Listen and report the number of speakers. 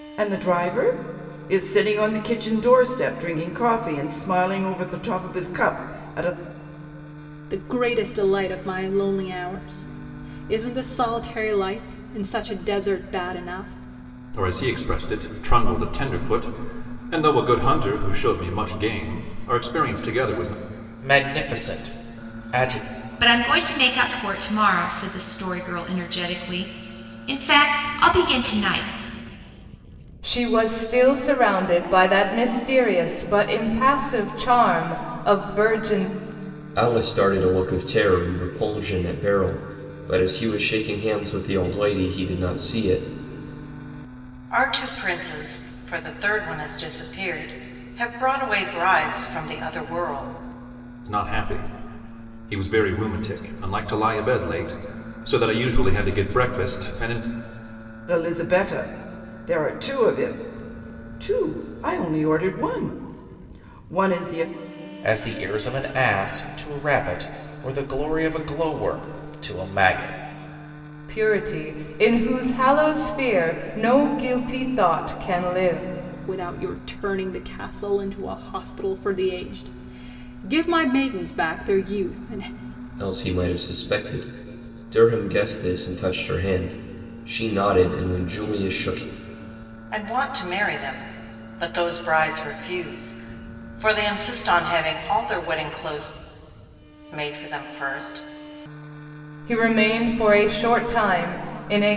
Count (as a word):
eight